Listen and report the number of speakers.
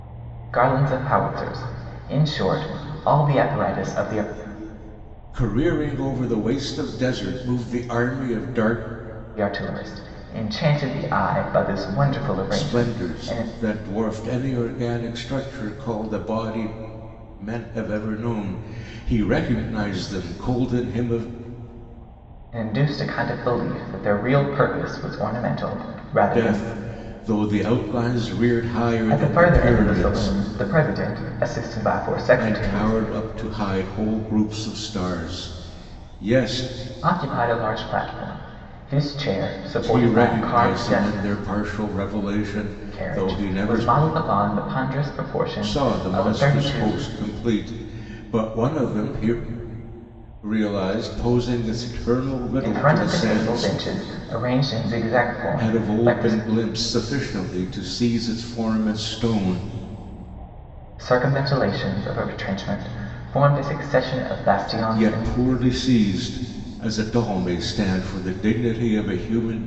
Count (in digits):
2